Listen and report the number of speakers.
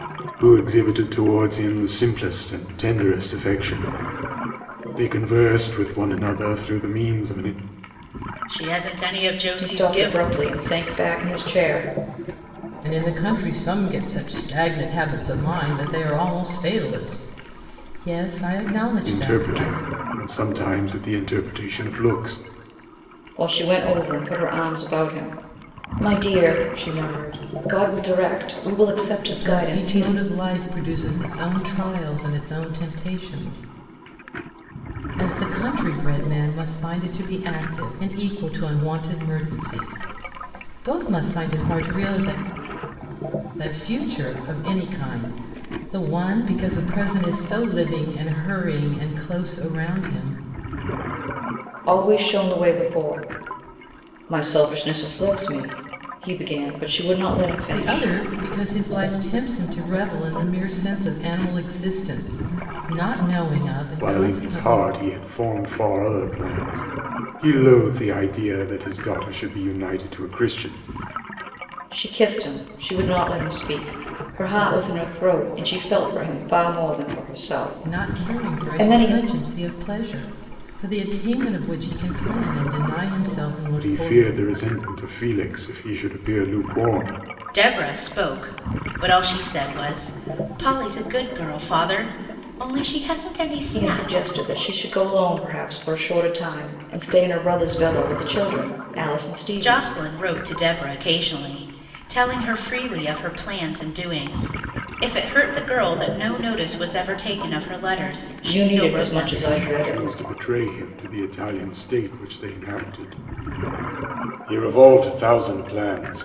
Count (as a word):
four